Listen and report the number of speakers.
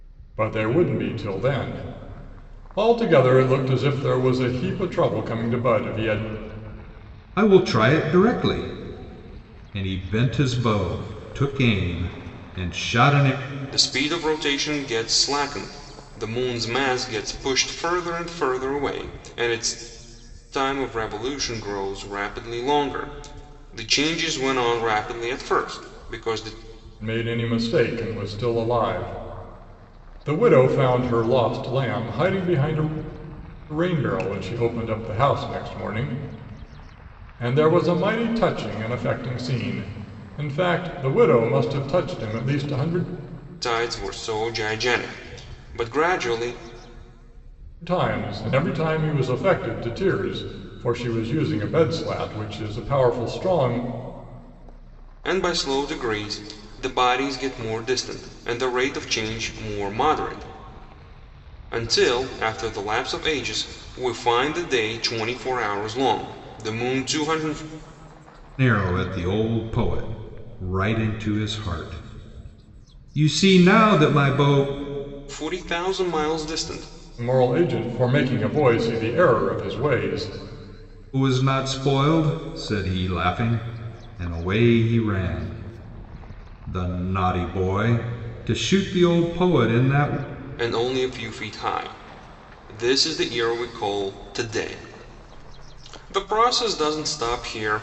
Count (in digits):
3